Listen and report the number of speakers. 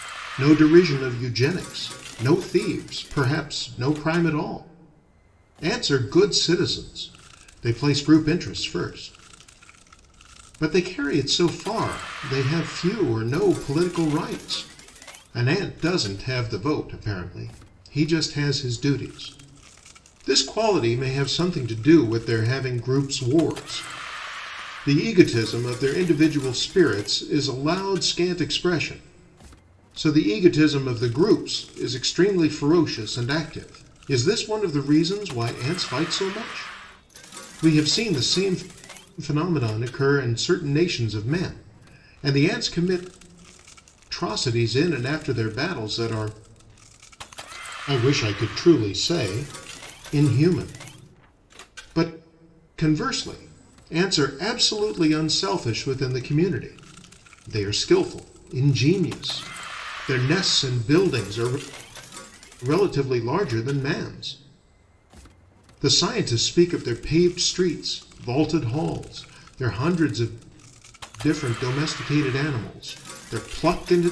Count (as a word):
one